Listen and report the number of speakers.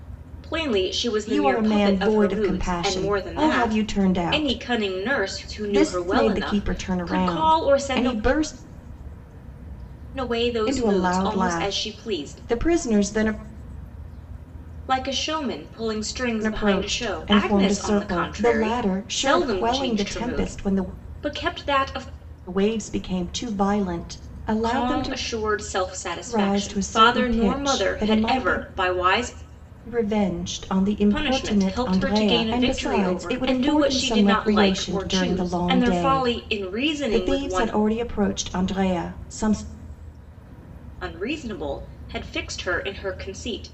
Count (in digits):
2